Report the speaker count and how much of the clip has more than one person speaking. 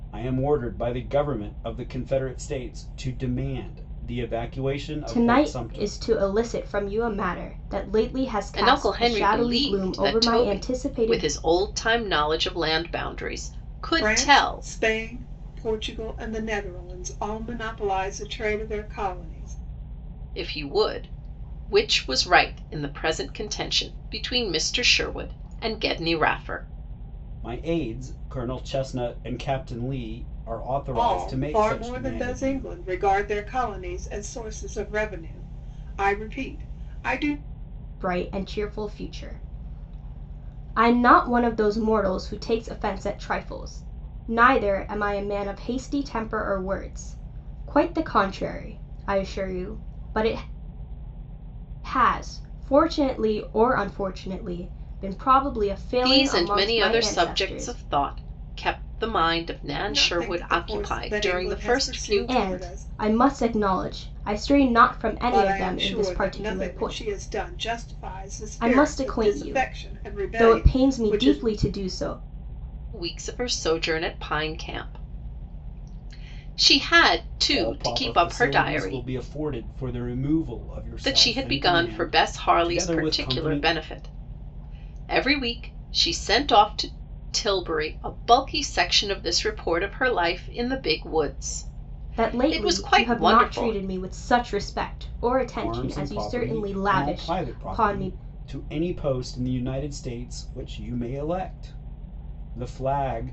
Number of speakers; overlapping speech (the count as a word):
four, about 24%